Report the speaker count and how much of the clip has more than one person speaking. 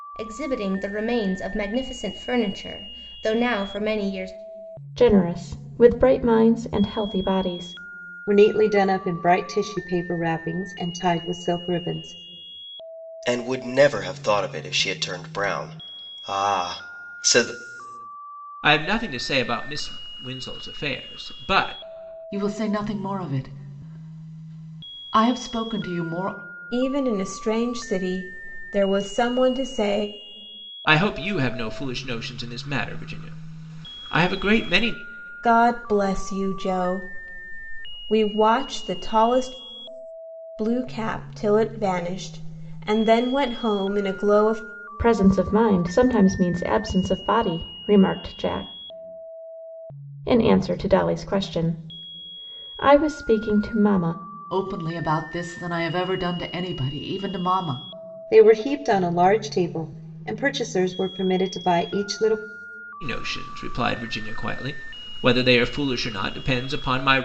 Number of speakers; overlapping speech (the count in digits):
7, no overlap